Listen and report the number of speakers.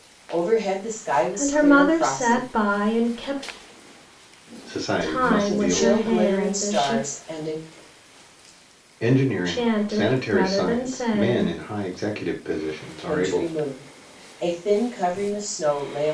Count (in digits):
3